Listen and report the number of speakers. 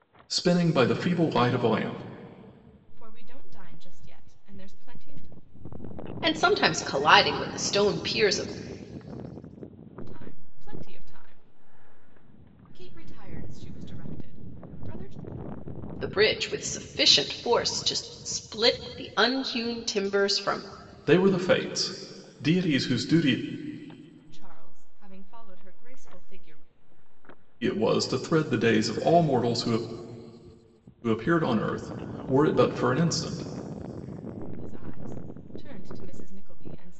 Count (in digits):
3